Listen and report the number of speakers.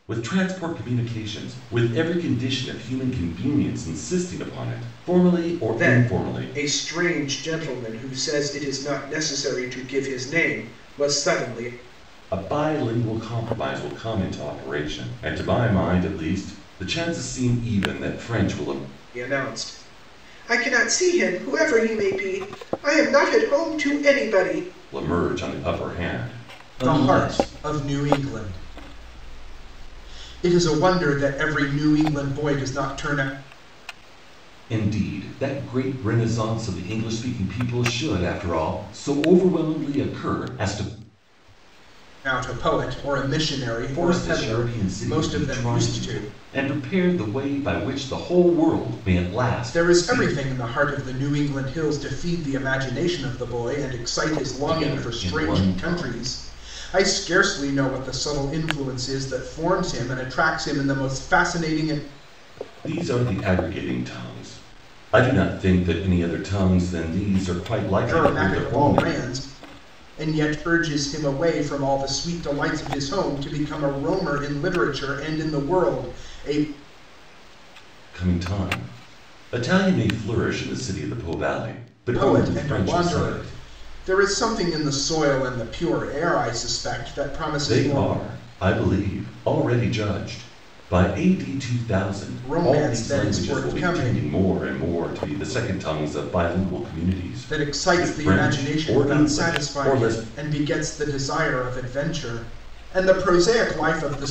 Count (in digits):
2